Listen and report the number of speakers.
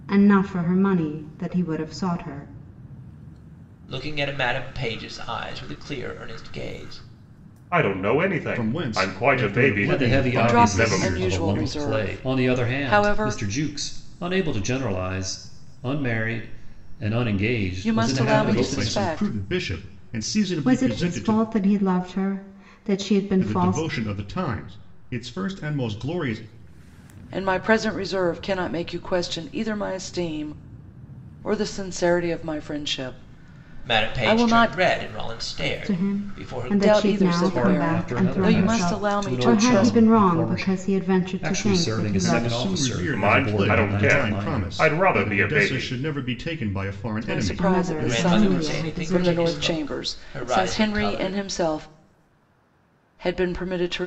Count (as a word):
six